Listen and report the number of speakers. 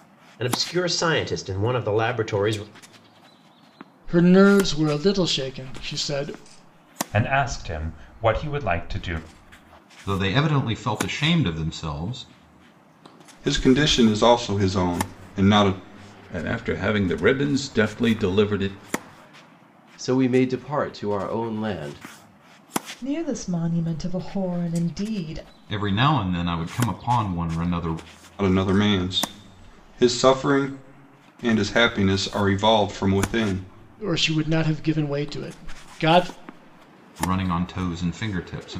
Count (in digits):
8